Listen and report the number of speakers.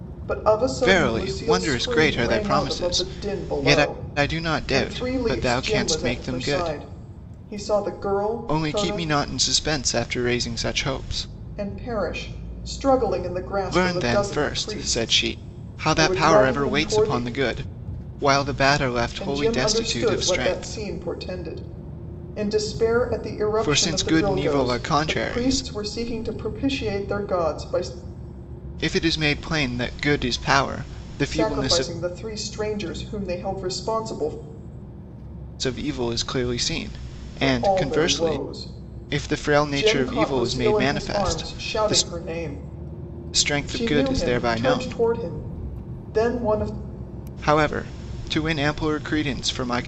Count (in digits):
2